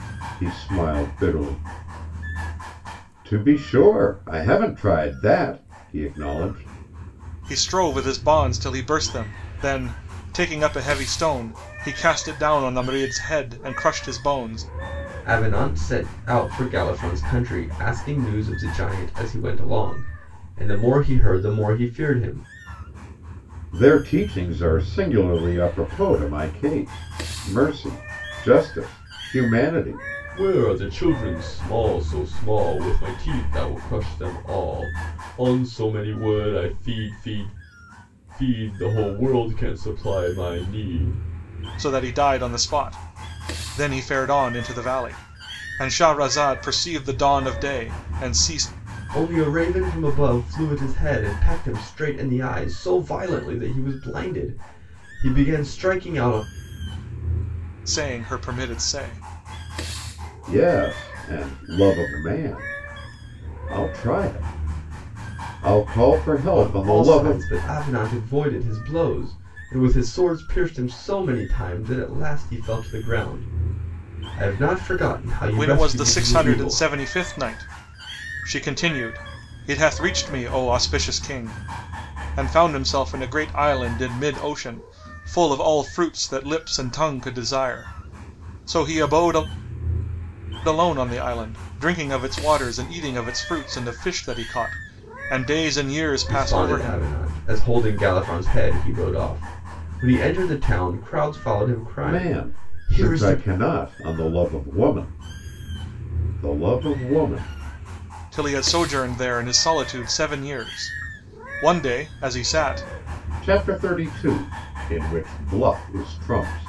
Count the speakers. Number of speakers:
3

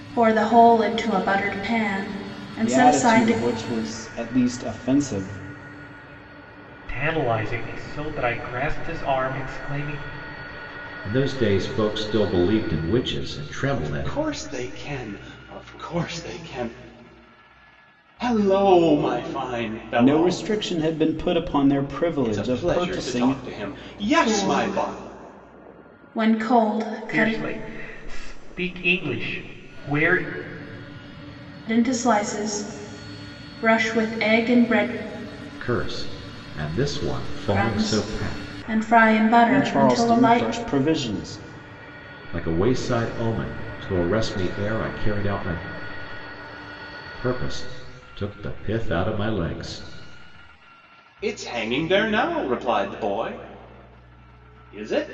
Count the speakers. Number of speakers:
5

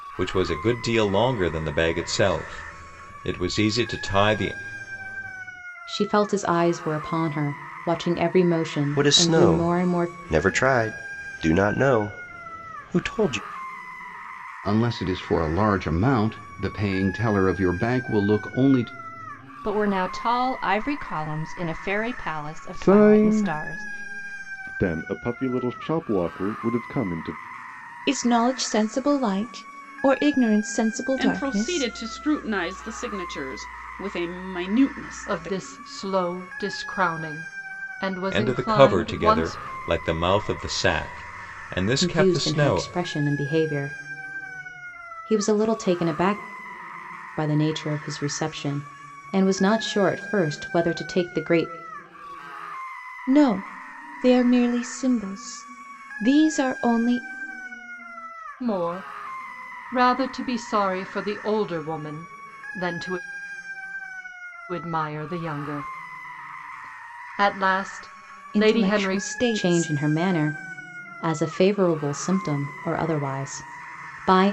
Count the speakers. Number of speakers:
9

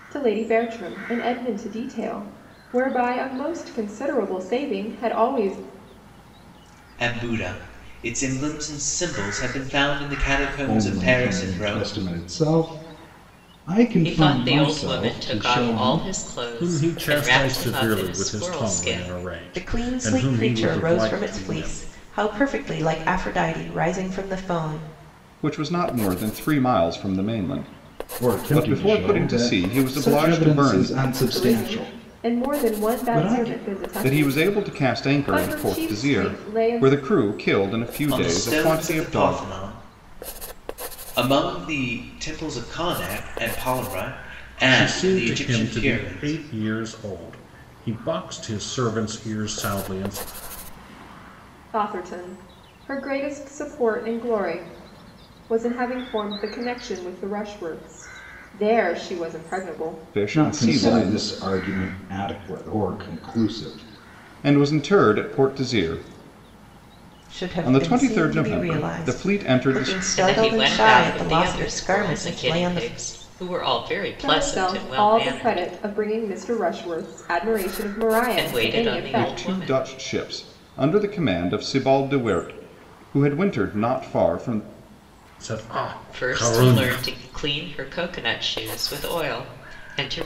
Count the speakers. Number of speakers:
7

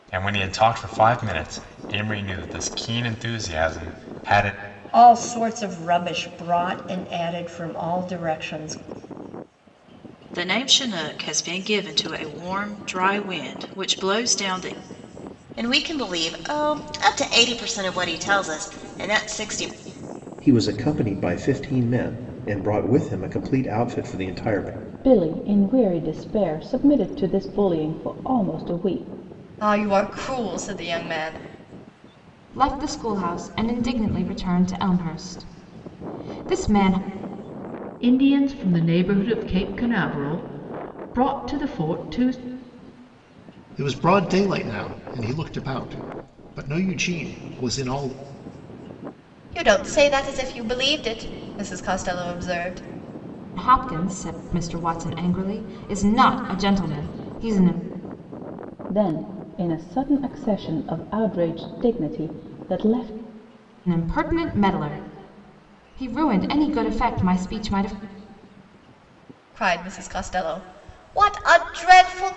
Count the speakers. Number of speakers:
10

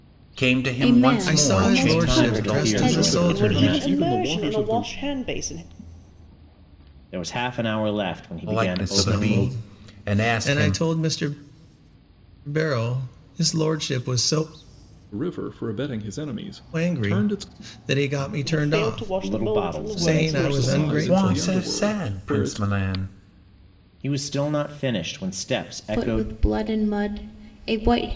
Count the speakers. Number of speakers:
6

